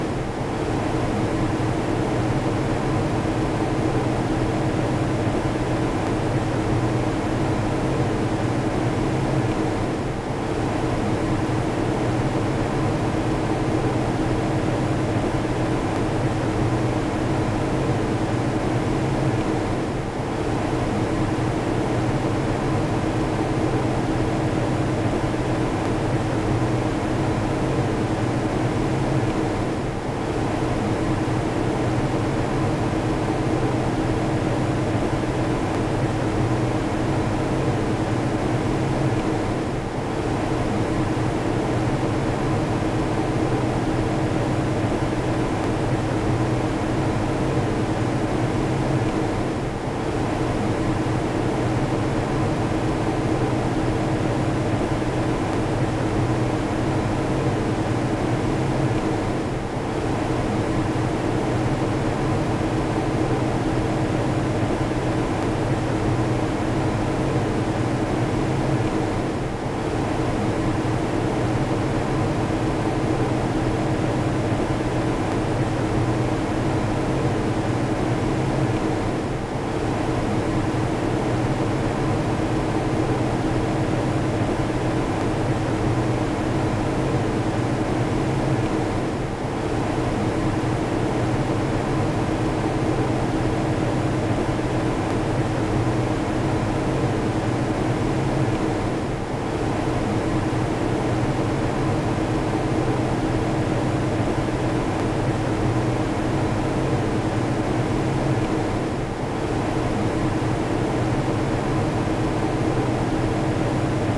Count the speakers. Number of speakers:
zero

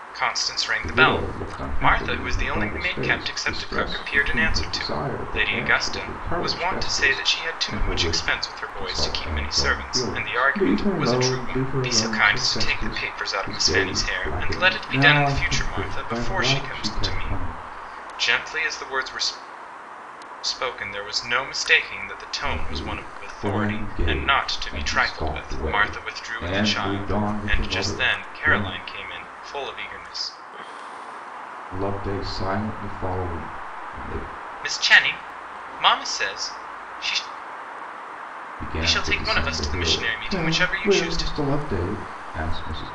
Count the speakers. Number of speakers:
two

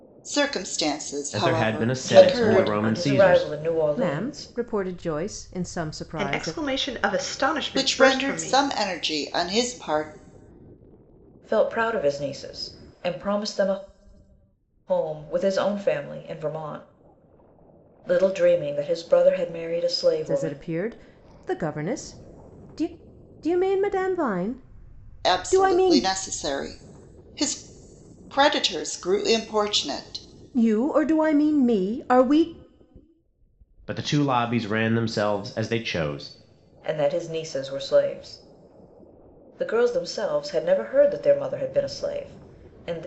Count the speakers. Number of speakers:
five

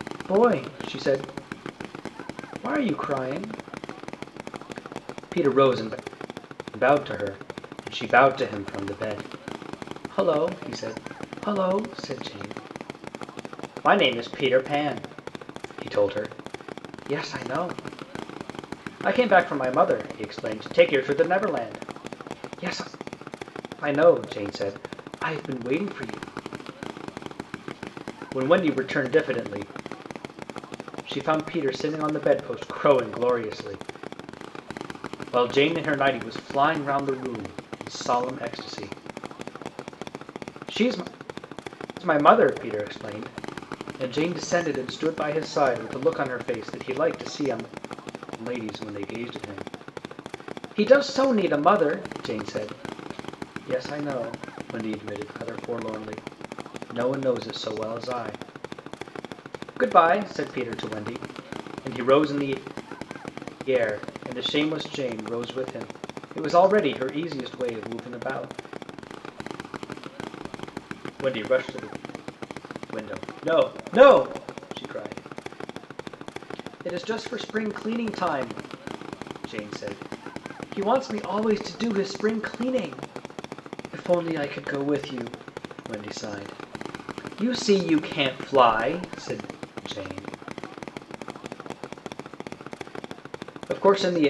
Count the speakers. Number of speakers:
one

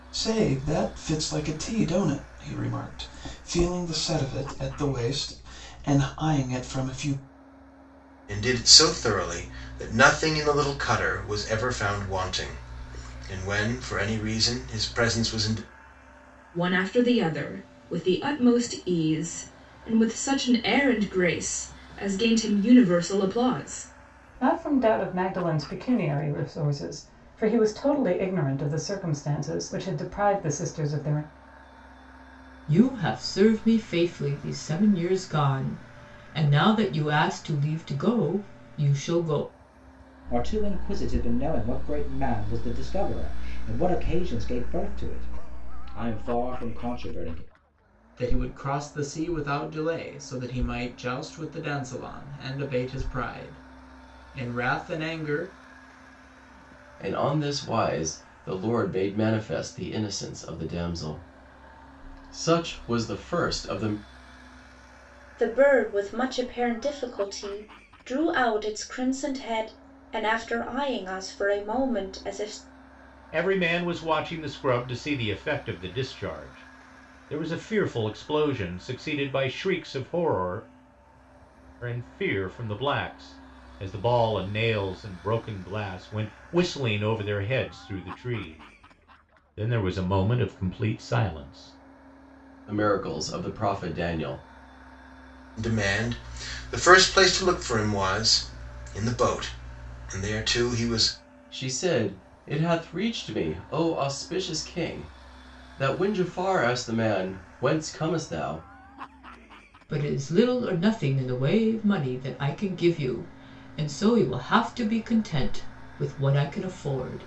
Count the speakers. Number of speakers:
ten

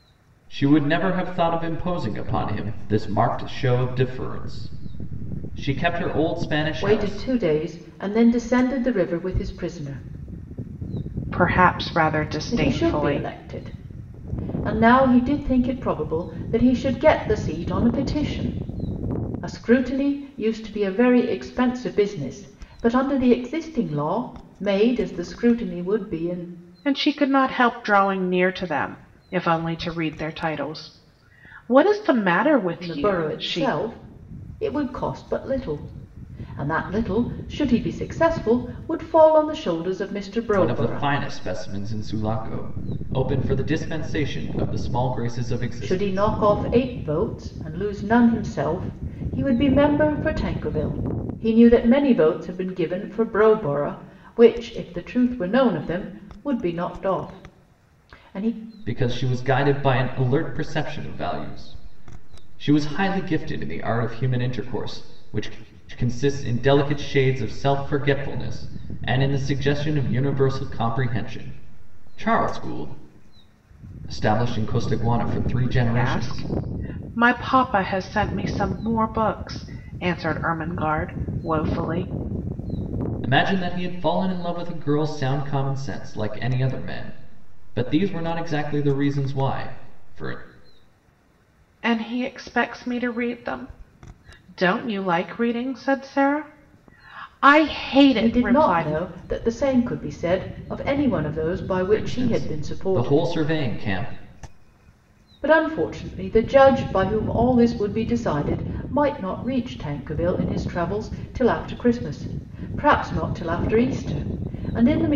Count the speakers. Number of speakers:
three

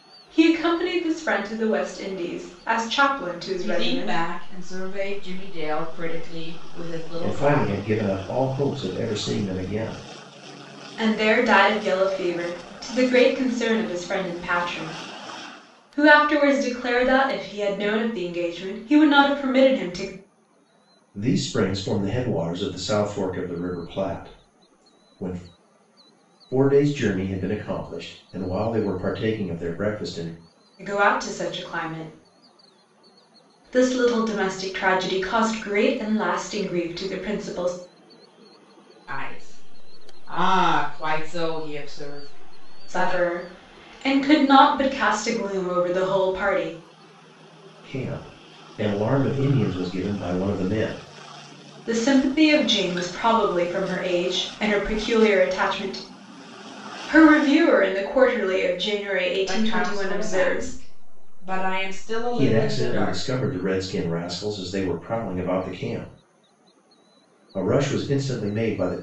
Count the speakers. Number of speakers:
three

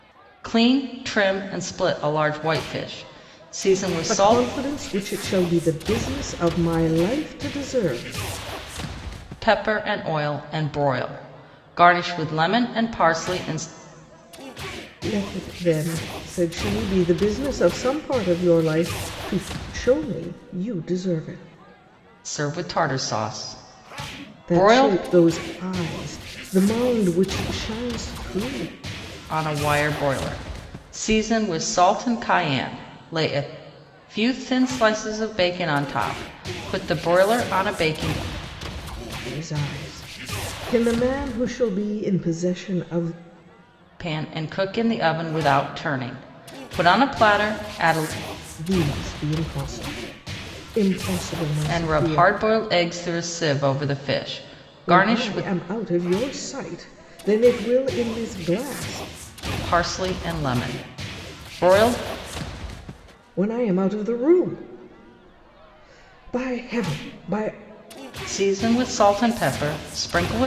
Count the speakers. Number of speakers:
two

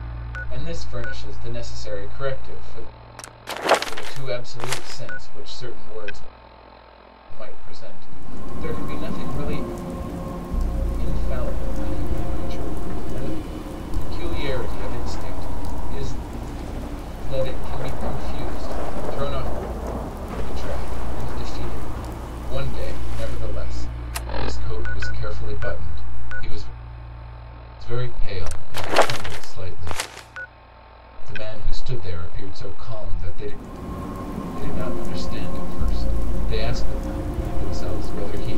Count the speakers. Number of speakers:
one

